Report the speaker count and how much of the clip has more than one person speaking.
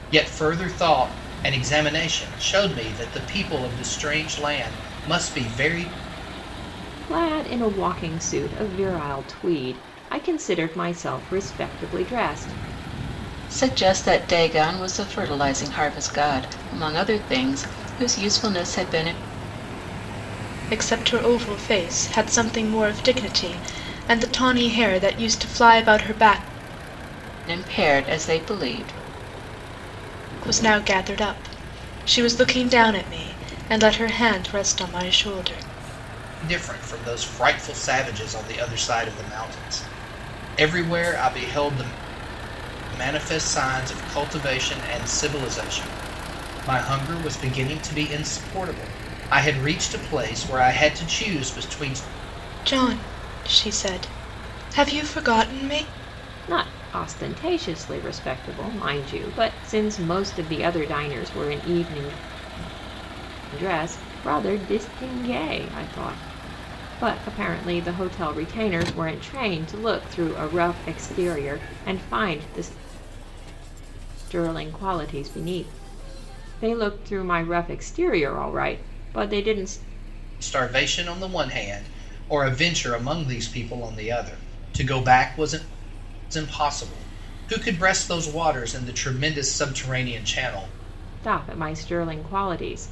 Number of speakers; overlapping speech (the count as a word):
four, no overlap